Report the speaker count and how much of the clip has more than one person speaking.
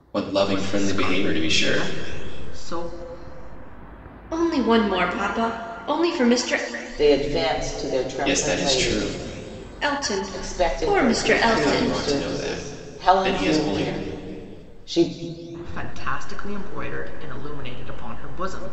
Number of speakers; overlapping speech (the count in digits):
4, about 30%